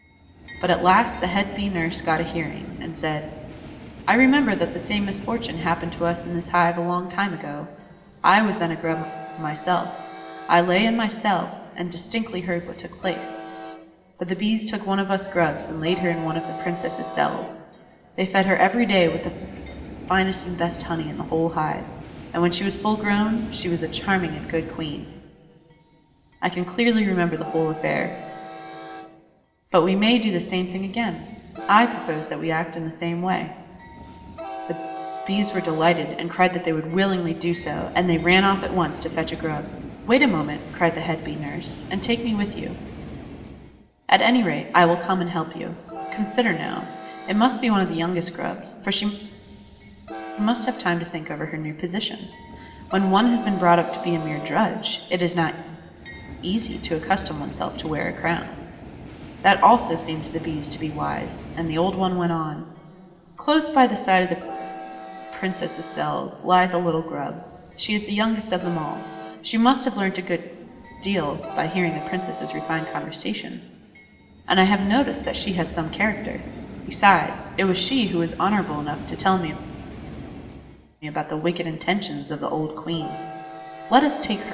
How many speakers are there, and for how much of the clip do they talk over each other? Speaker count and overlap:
1, no overlap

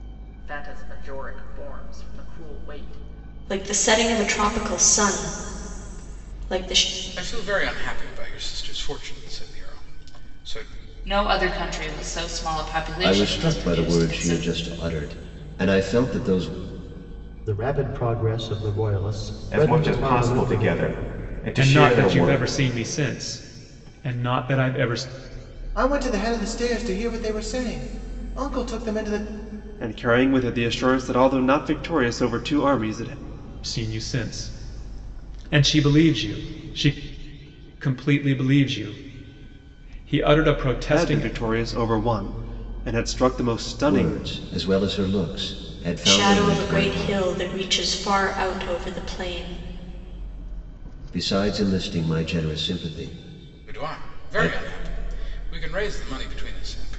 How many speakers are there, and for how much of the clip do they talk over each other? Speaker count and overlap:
10, about 12%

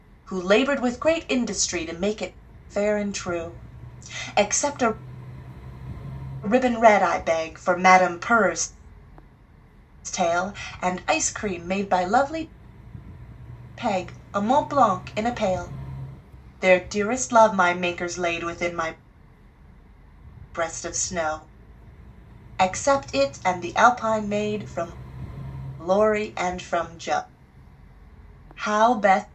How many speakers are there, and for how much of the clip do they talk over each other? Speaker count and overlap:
1, no overlap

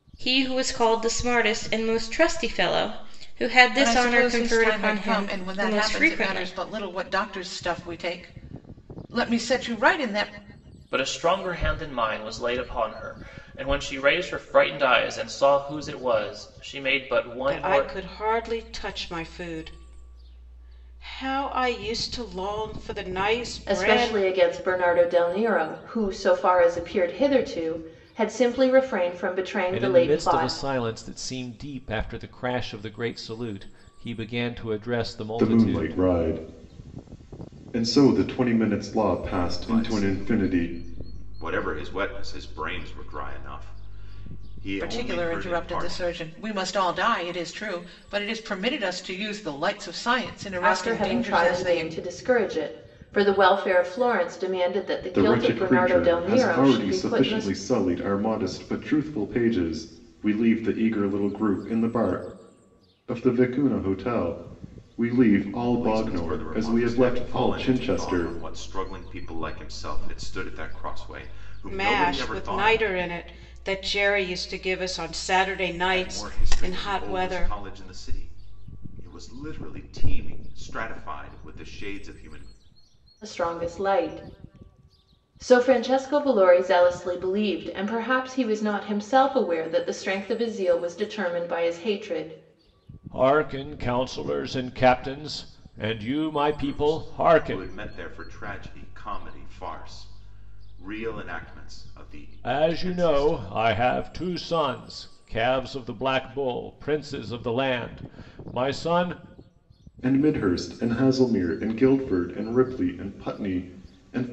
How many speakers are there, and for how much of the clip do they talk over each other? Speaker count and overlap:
8, about 17%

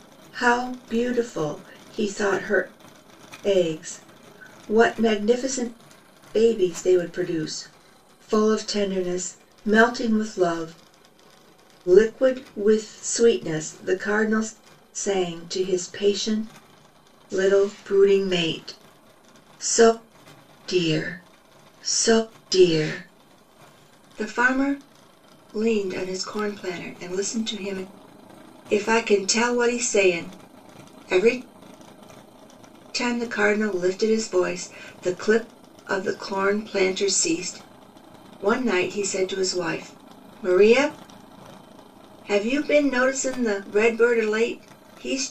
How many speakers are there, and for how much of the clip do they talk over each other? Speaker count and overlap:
1, no overlap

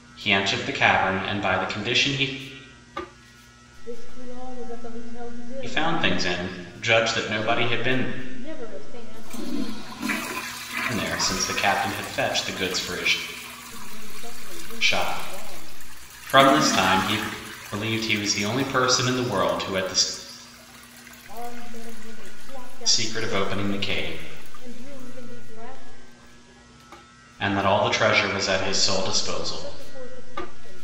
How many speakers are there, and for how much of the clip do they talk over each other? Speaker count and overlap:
2, about 16%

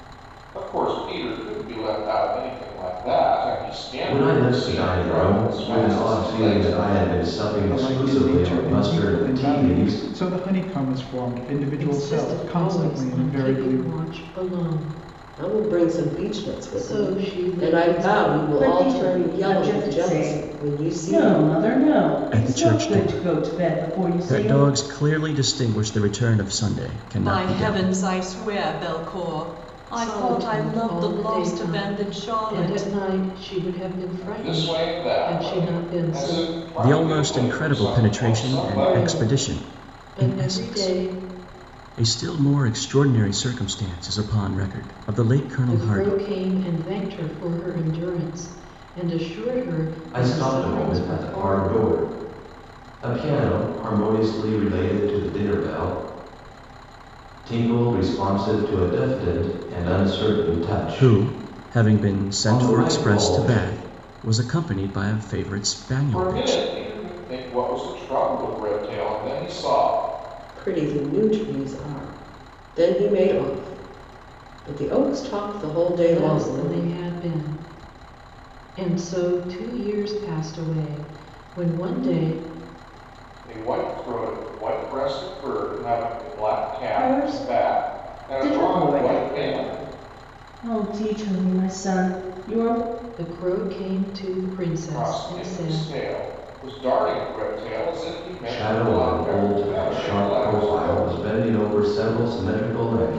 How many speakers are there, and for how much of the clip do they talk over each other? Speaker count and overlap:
8, about 37%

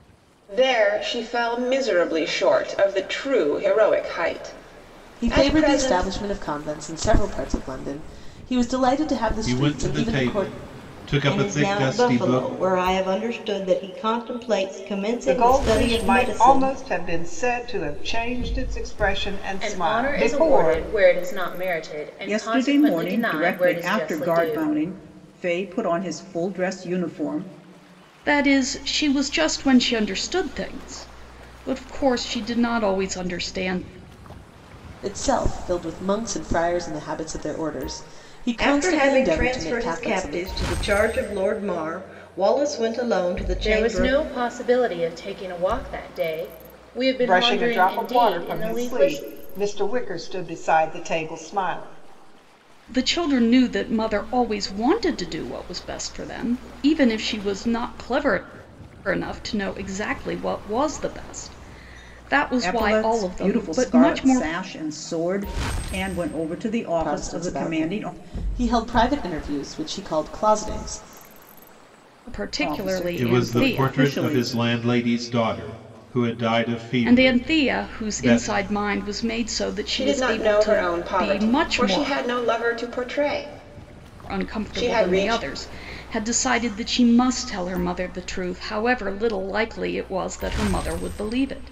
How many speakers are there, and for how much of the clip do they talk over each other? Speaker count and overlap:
8, about 25%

